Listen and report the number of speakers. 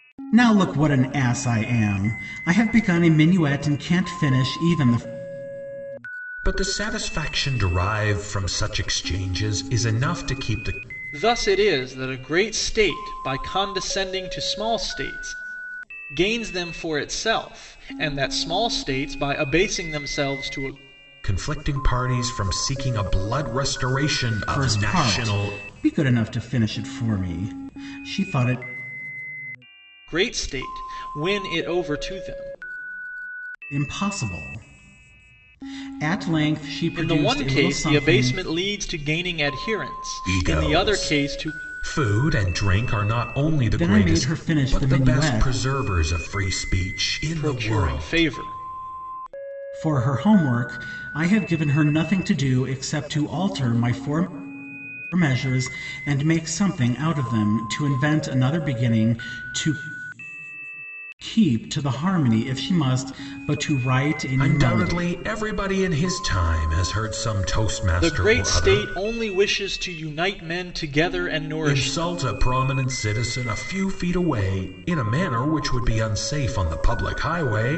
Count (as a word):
three